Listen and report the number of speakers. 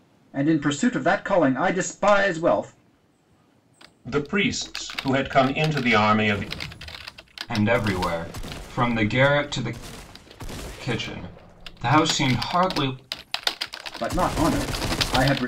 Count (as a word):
three